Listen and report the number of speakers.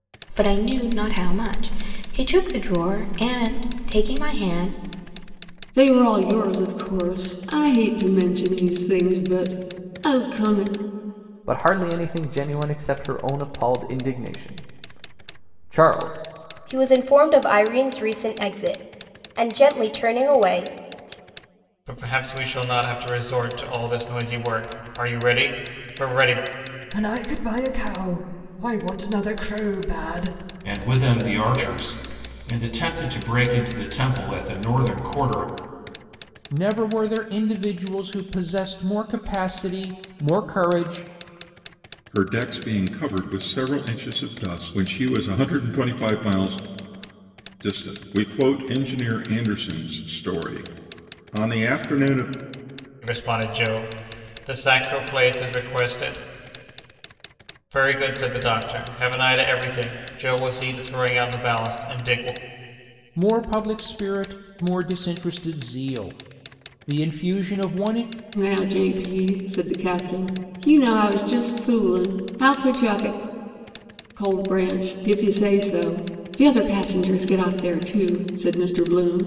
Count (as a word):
nine